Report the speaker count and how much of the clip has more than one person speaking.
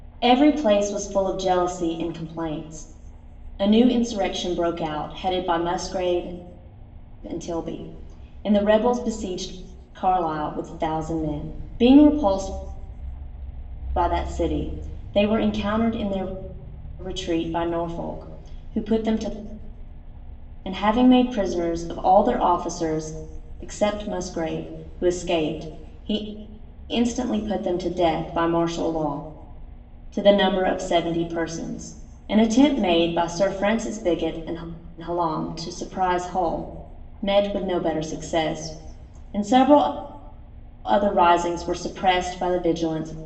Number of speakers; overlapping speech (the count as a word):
one, no overlap